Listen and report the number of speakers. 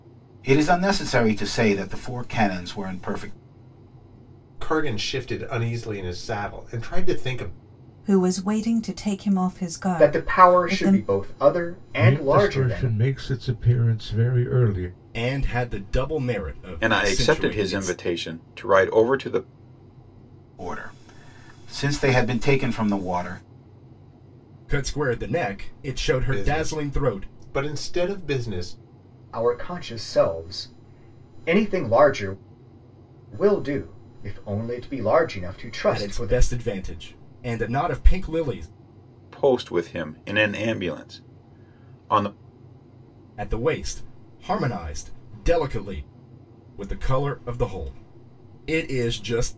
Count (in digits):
7